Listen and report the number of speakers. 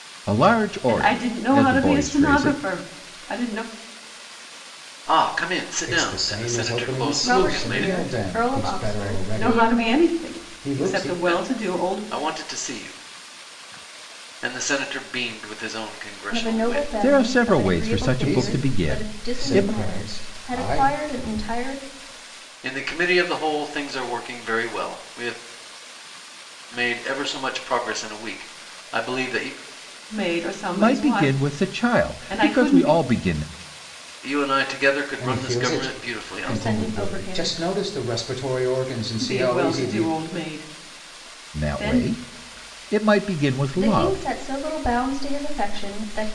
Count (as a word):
five